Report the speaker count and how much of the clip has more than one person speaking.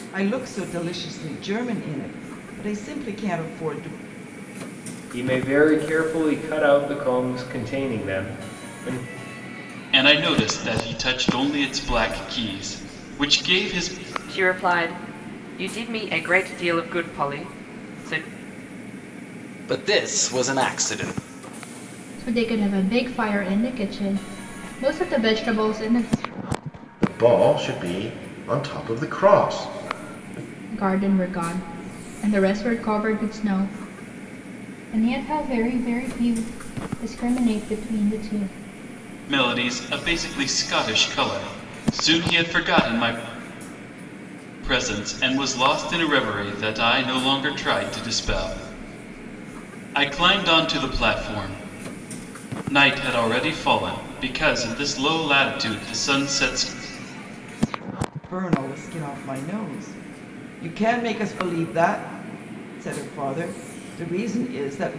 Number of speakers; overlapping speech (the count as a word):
seven, no overlap